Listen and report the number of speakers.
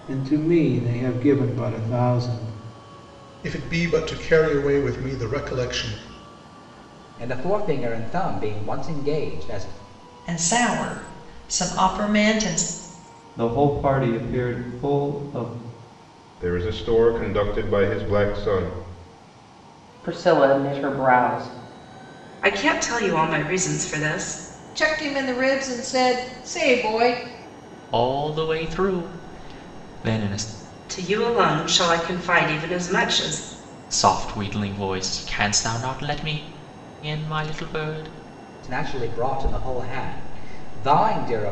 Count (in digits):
10